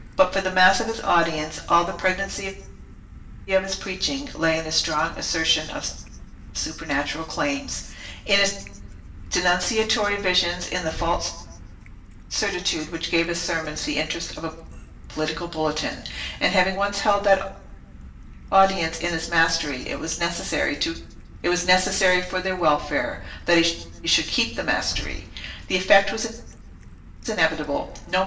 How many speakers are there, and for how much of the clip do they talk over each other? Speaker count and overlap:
1, no overlap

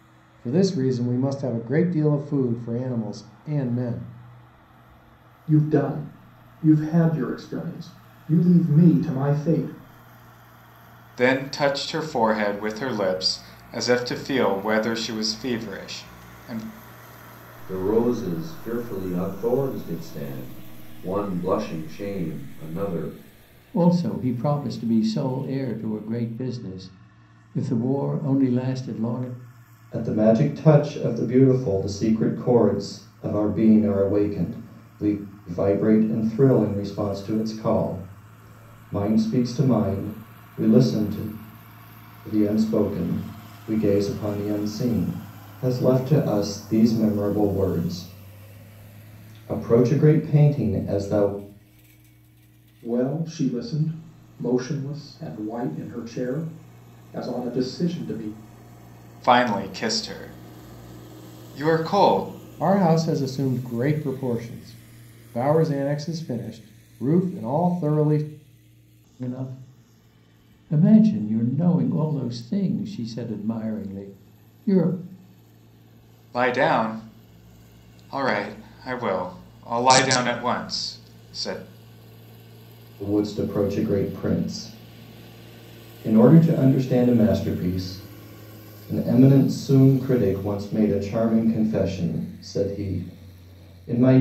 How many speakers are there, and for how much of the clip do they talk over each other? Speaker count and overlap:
6, no overlap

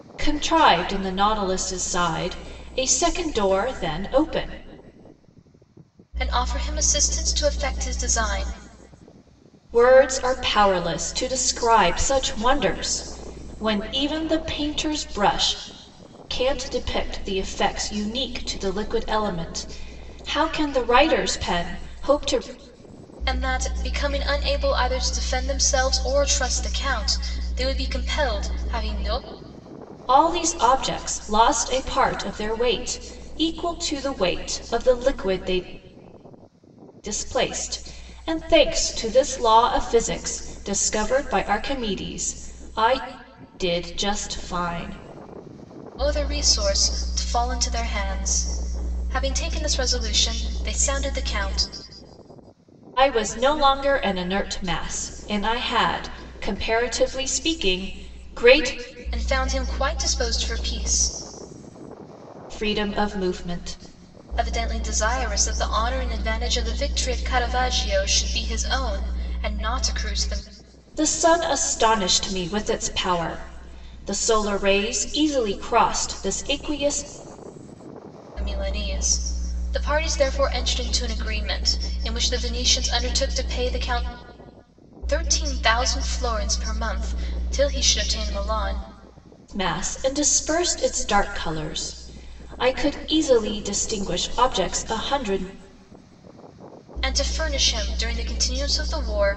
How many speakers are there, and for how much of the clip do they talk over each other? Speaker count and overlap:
2, no overlap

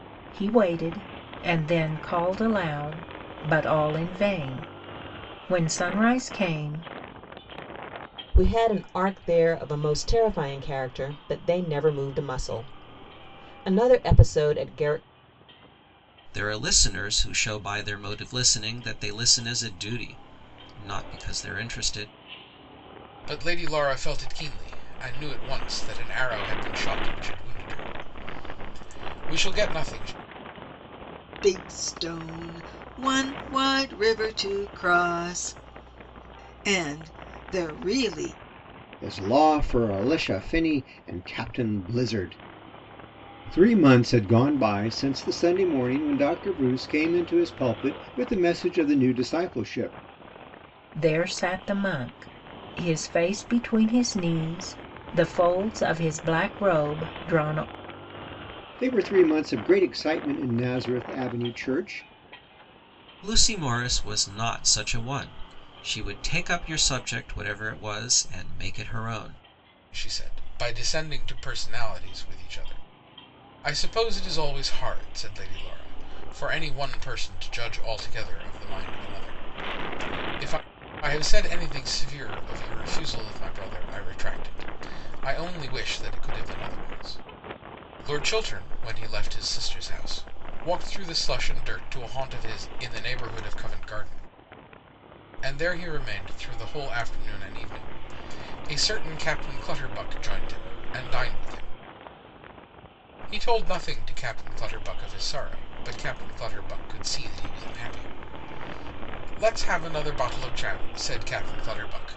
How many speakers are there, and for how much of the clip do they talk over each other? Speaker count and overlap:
6, no overlap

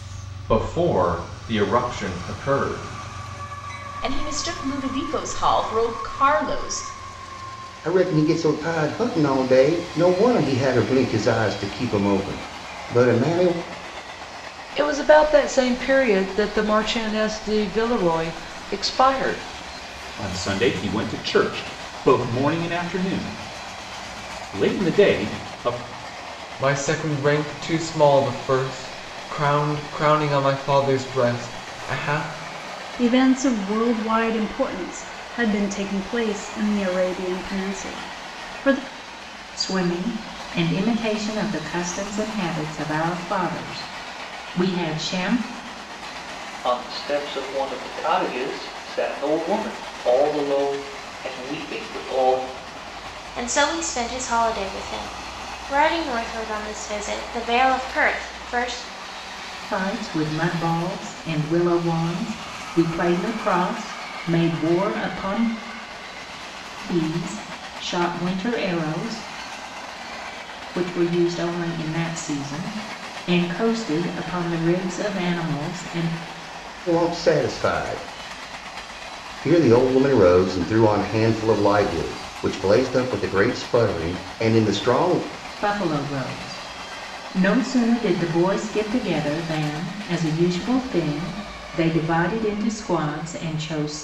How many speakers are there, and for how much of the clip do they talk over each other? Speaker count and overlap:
10, no overlap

